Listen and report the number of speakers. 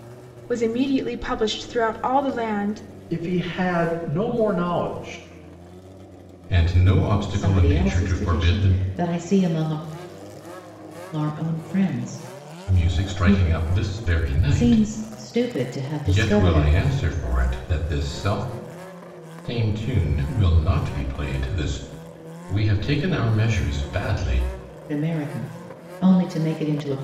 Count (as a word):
four